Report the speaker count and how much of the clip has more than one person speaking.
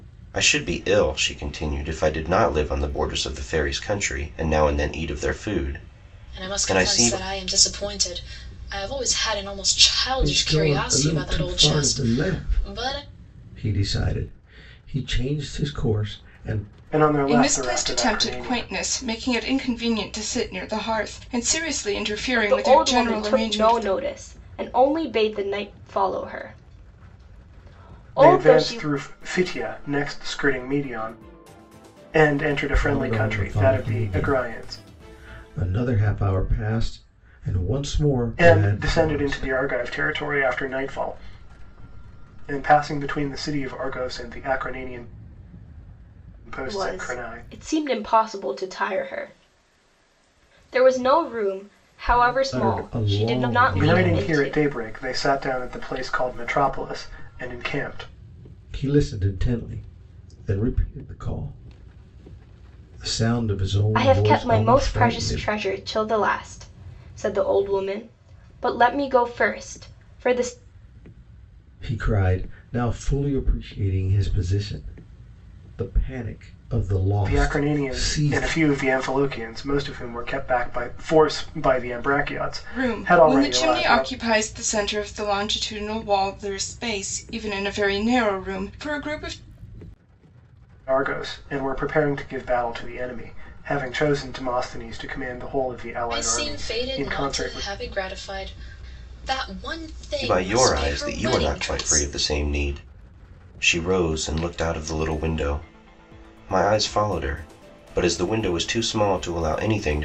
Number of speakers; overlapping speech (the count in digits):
6, about 20%